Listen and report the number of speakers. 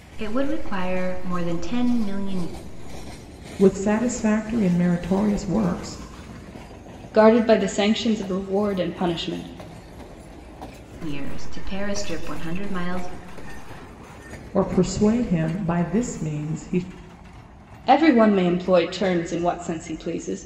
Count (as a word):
three